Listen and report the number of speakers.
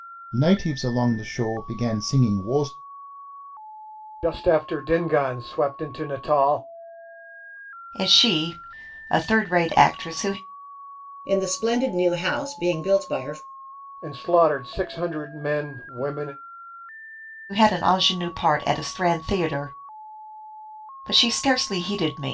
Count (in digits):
4